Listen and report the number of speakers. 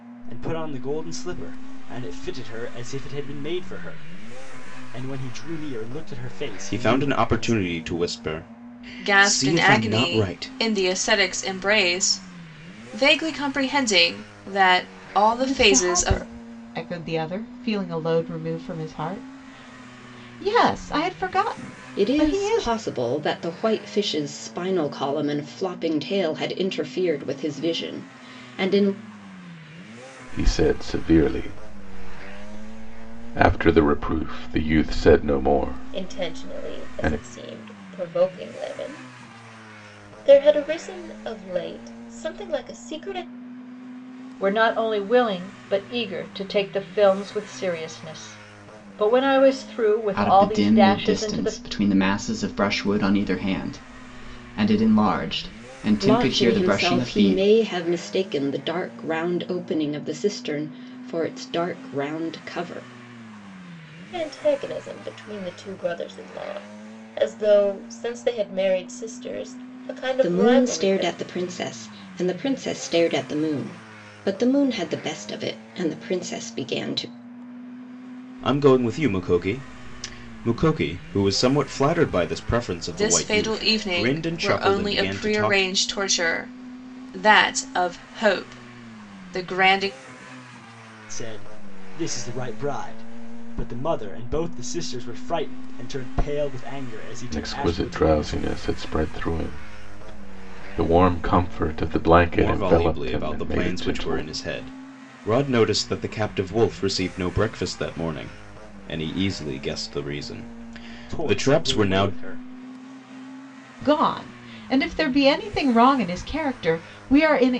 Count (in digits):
9